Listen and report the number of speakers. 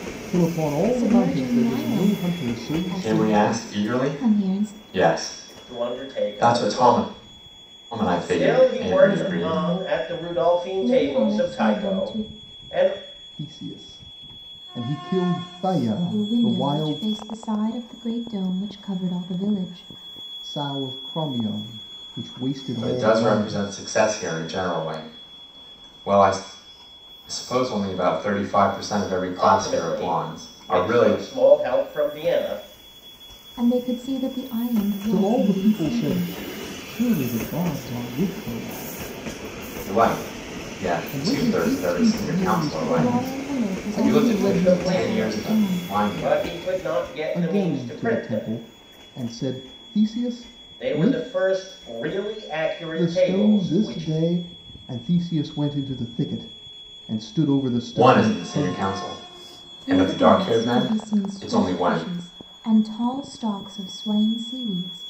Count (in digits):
4